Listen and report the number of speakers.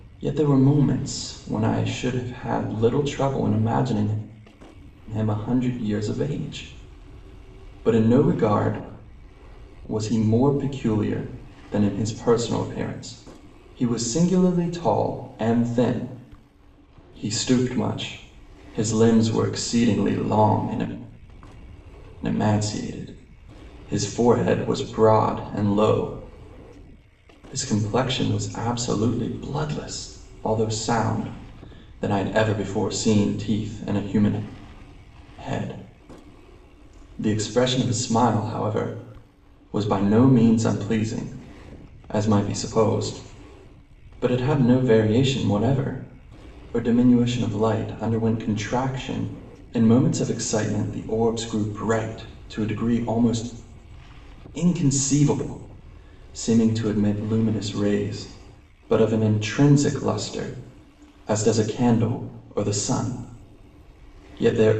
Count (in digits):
1